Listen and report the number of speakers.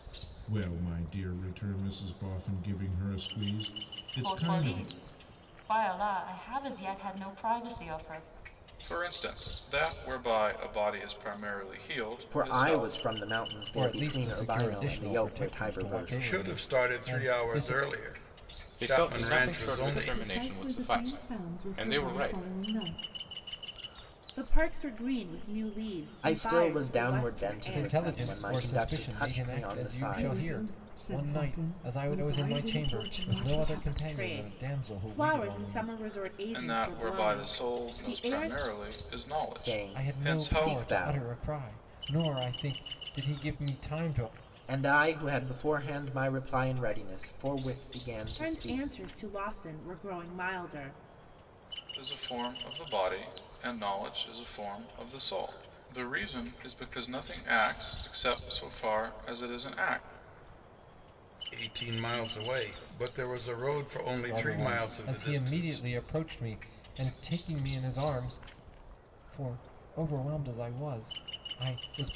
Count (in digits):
9